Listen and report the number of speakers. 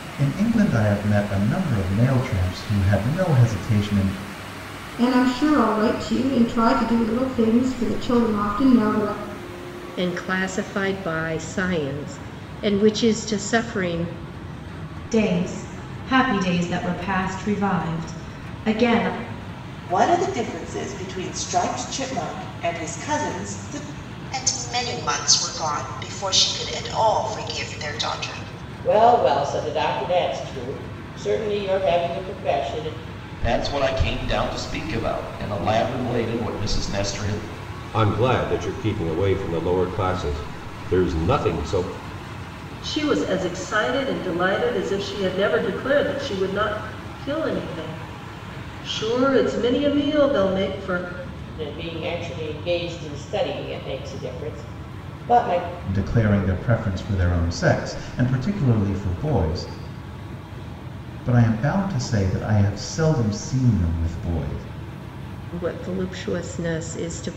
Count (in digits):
10